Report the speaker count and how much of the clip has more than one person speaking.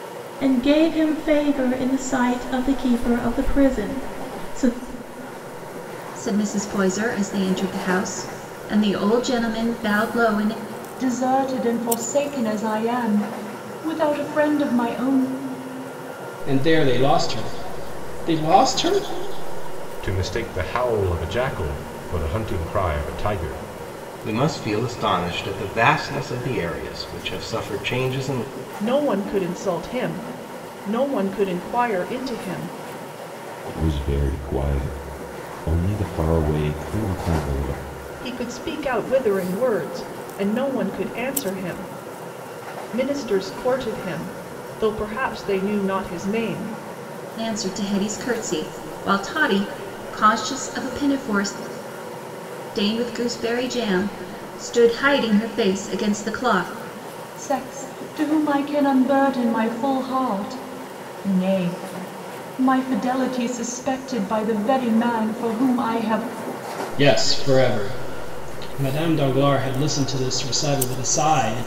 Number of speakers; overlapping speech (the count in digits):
8, no overlap